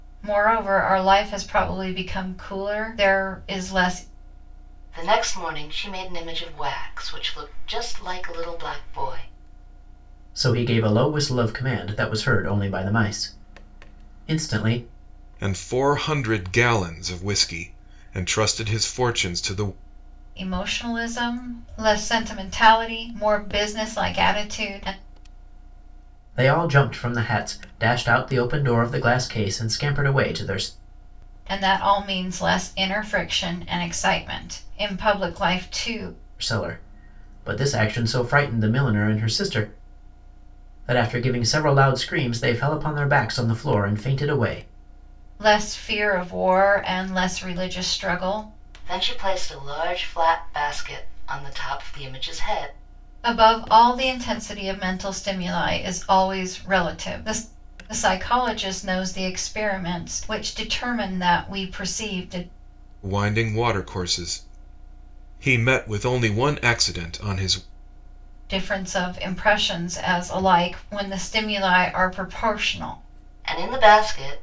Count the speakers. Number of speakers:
4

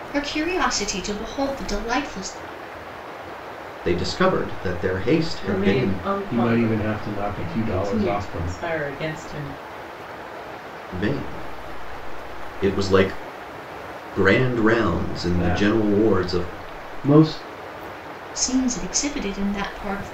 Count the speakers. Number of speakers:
4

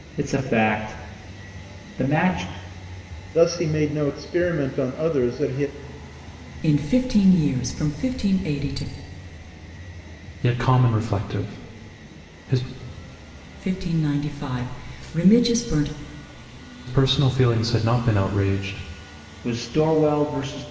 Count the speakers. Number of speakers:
4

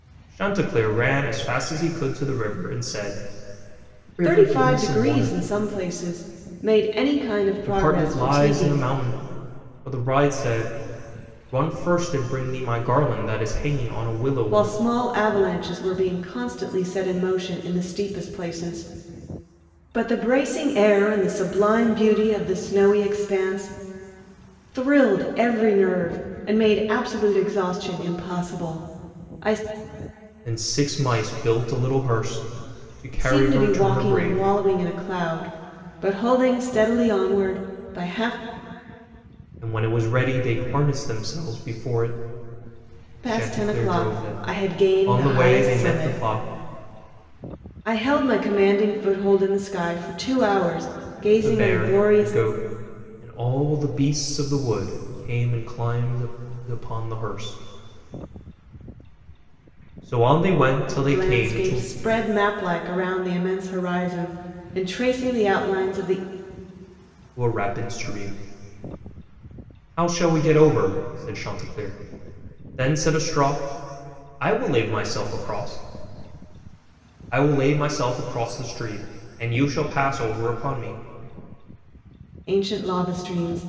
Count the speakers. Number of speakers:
2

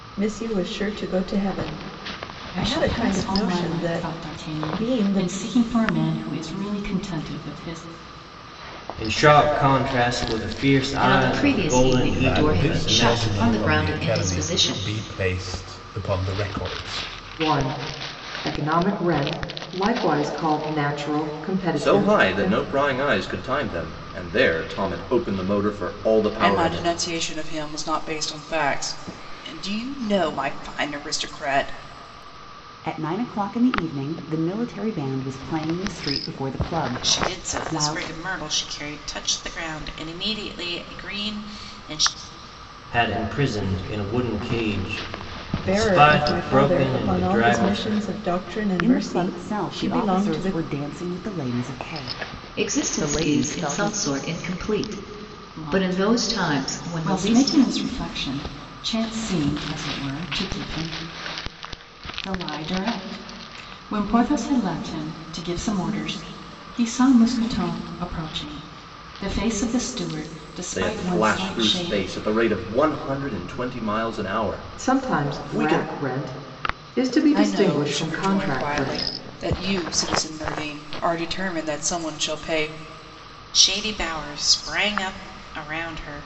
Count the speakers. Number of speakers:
10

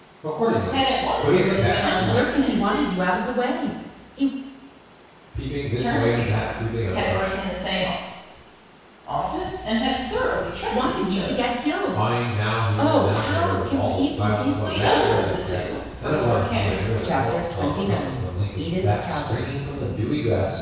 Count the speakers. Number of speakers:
3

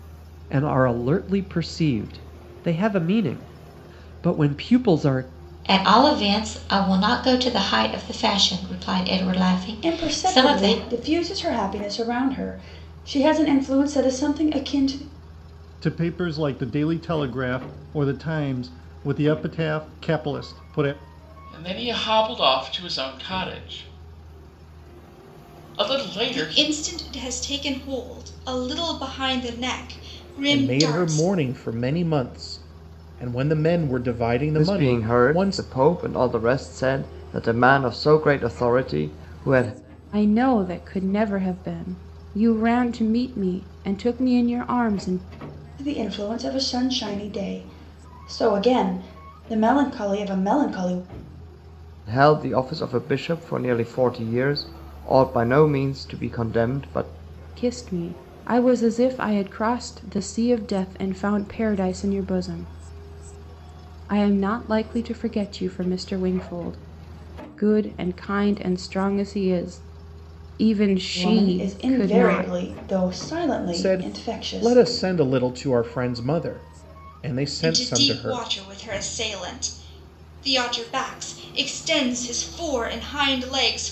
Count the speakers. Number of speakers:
9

